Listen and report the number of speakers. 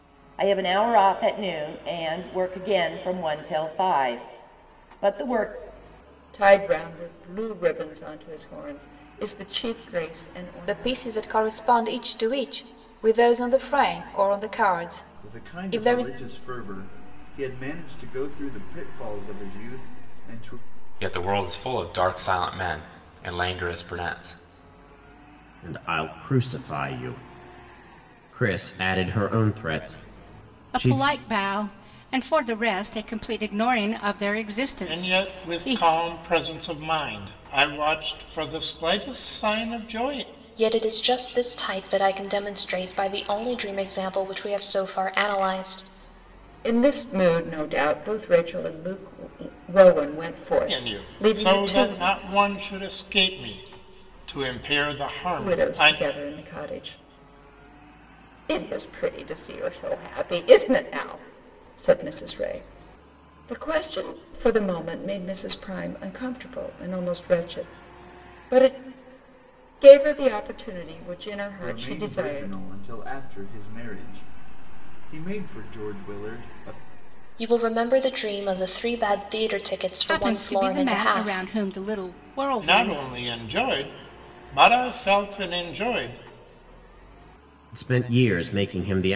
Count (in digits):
9